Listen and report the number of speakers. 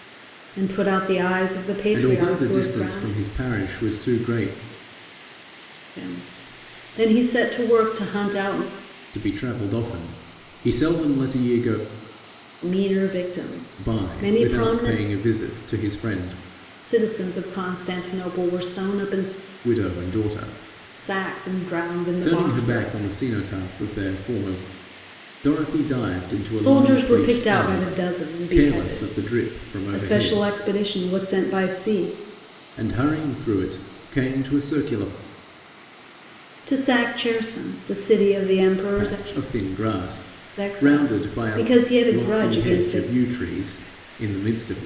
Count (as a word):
two